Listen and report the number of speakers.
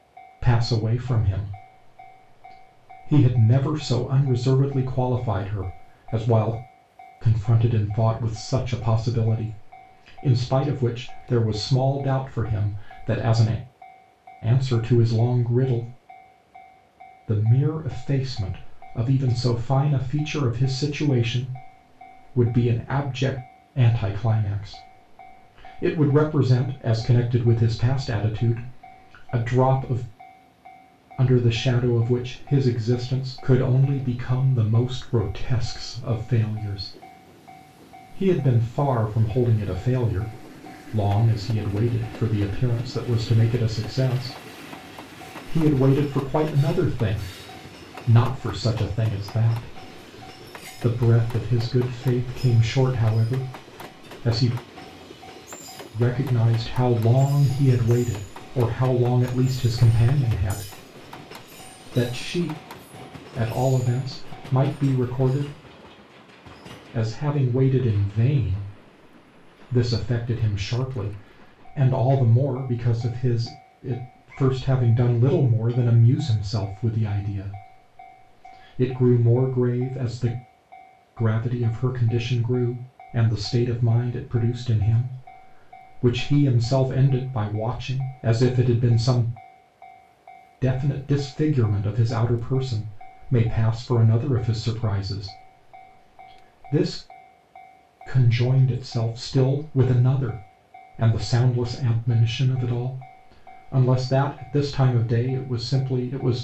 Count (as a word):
one